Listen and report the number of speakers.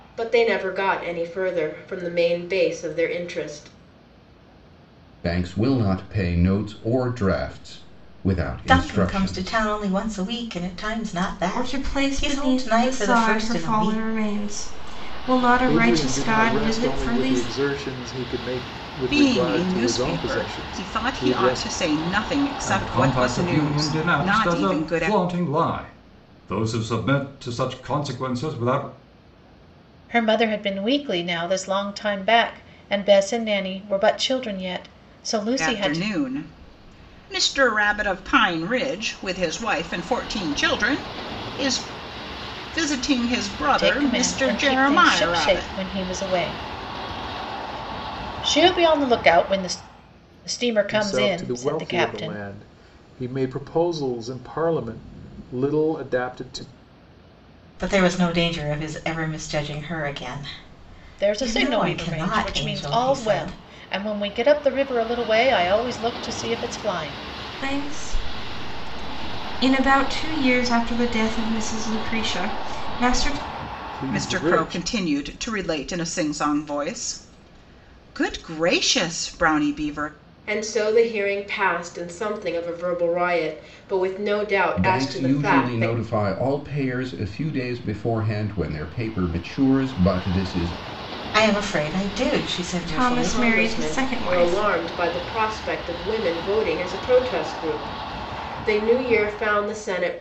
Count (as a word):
eight